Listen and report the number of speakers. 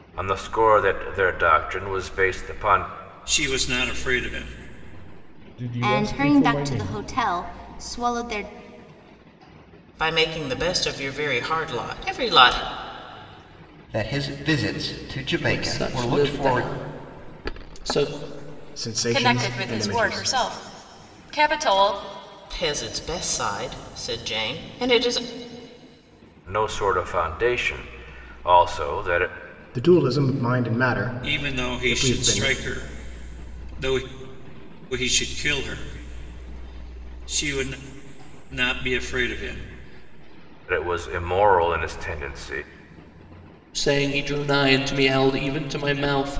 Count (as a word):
nine